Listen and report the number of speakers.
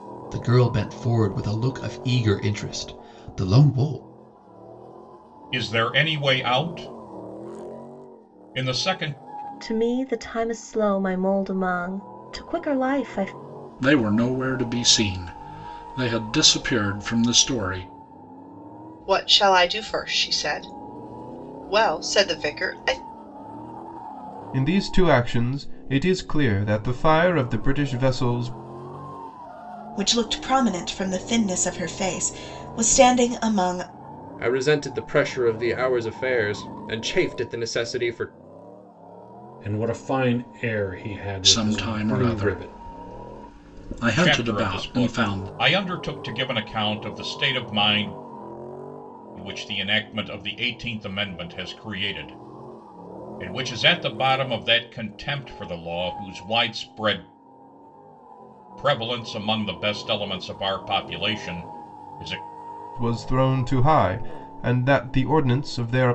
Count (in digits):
9